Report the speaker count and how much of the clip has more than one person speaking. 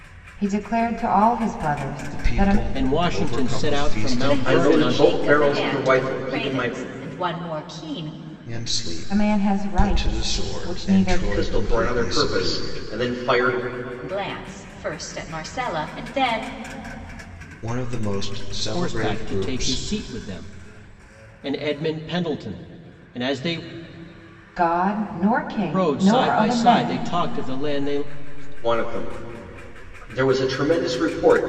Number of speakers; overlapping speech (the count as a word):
six, about 39%